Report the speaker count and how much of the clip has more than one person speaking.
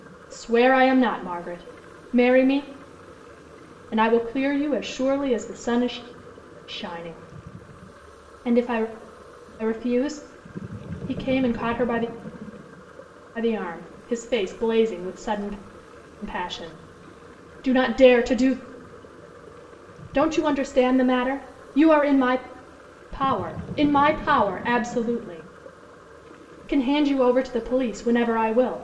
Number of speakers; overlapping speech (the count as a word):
one, no overlap